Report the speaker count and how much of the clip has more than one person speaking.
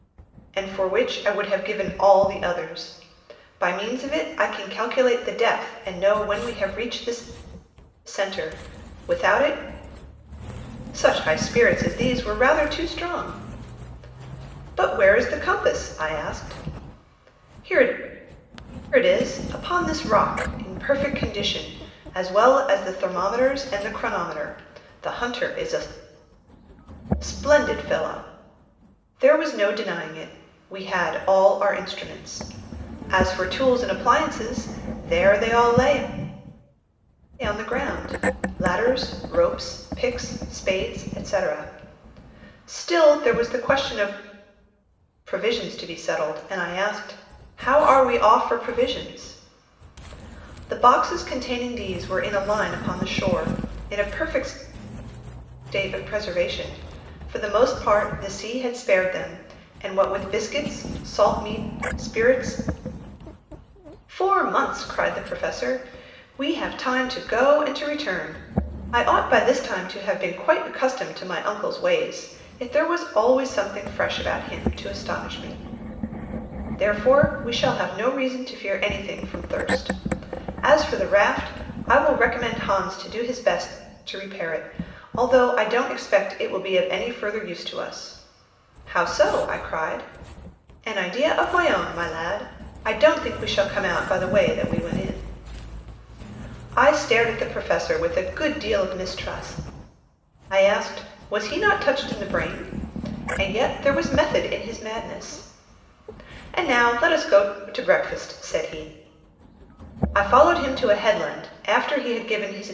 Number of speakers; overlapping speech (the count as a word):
one, no overlap